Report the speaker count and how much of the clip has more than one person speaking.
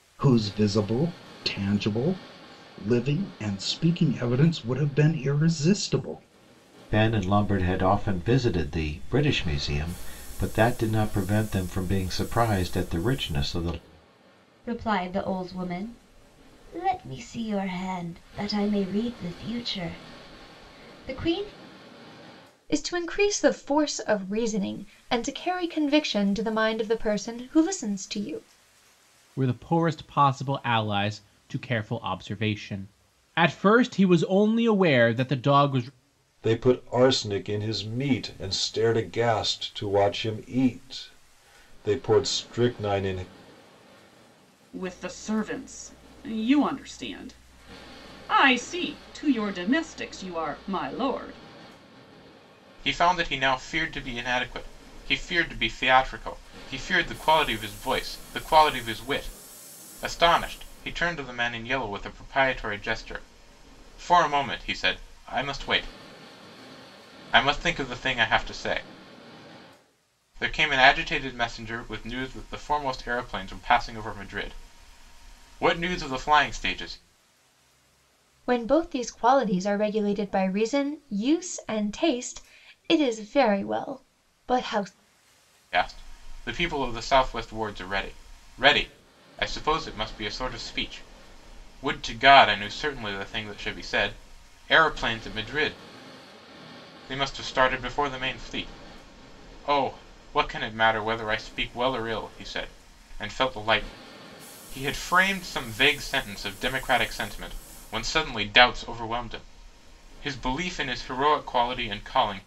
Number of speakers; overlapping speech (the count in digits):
8, no overlap